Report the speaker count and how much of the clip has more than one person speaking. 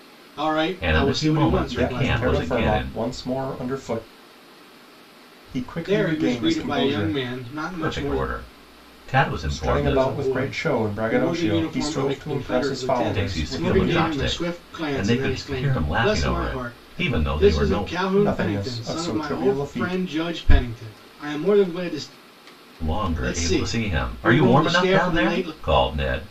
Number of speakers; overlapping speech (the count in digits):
3, about 63%